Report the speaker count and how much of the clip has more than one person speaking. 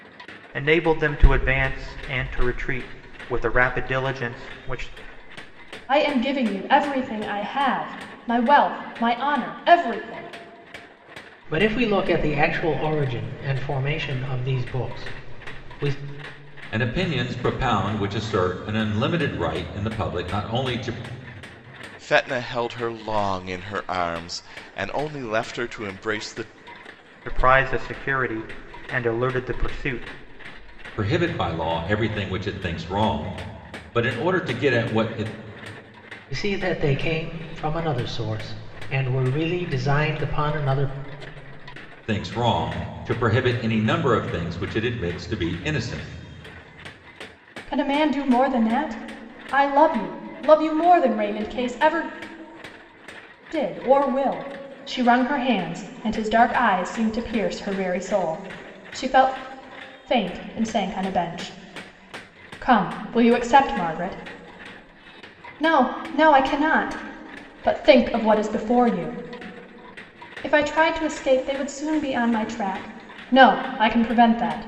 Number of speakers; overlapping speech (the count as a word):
five, no overlap